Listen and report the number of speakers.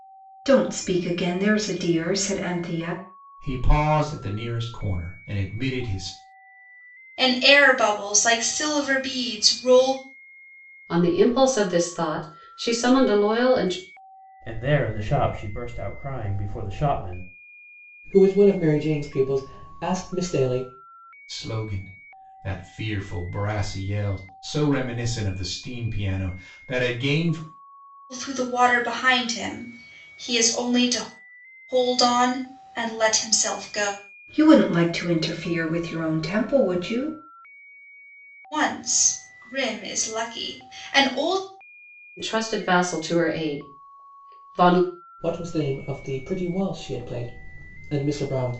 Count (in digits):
6